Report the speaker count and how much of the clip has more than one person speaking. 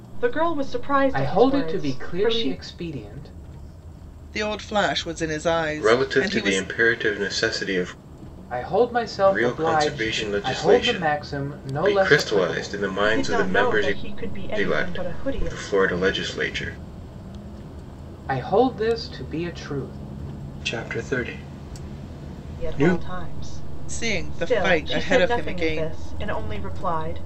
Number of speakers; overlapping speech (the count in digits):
4, about 35%